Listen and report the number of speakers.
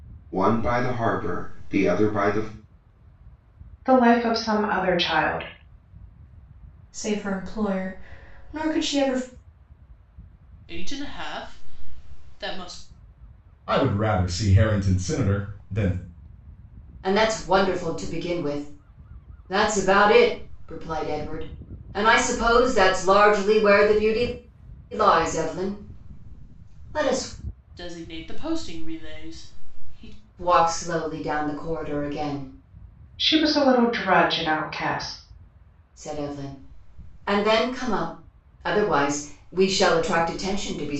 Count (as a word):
six